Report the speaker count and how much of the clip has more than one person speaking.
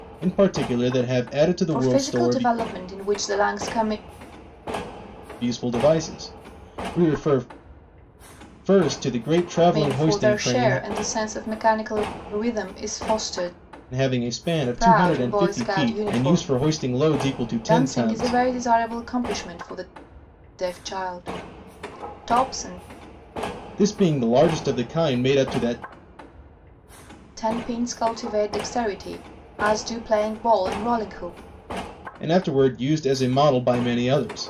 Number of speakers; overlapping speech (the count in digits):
2, about 13%